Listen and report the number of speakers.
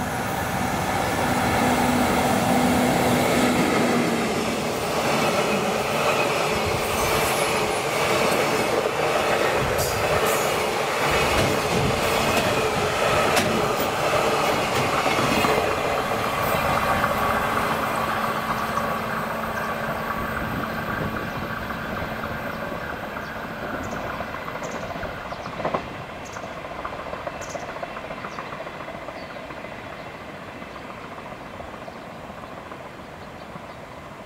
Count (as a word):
zero